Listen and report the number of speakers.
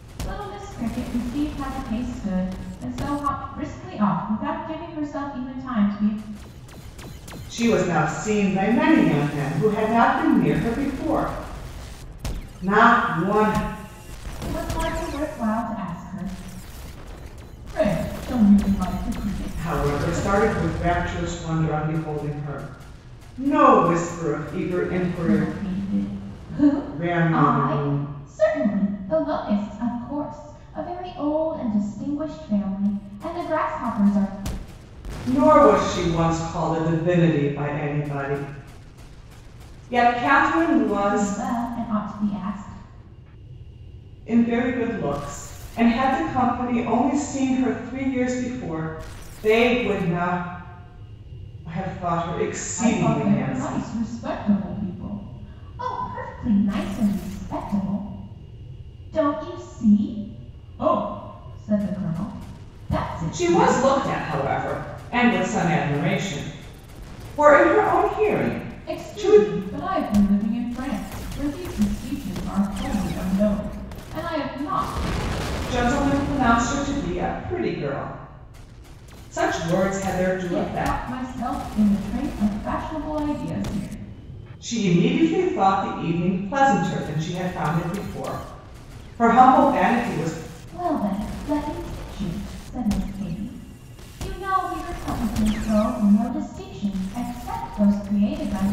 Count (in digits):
2